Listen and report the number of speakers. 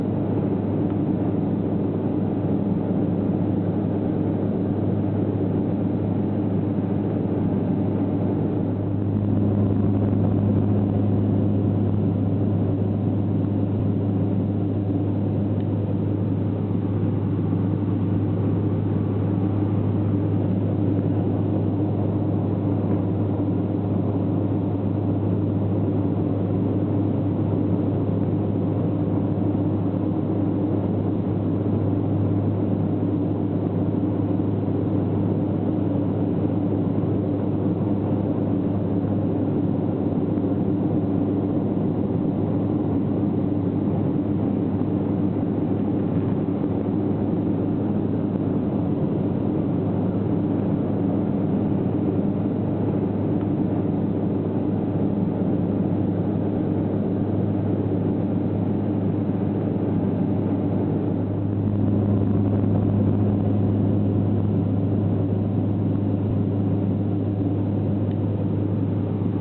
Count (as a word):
zero